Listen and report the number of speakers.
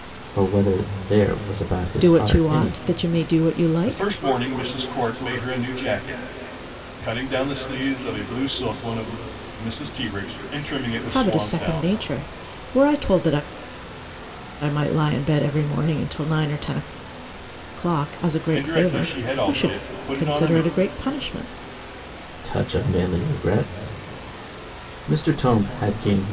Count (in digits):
3